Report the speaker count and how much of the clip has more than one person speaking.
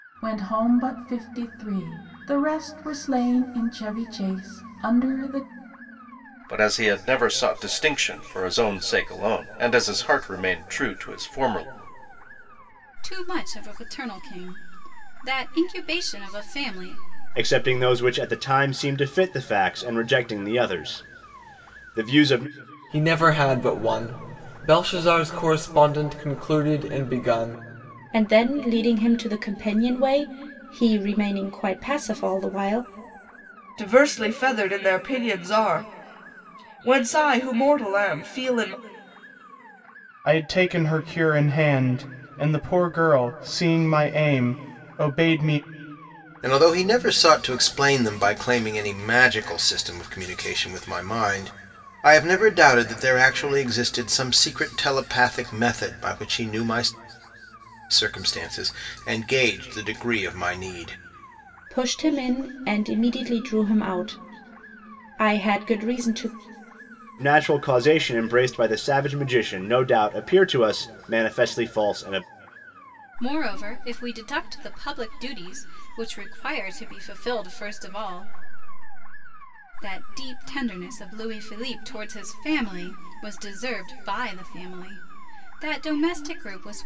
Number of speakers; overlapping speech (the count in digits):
9, no overlap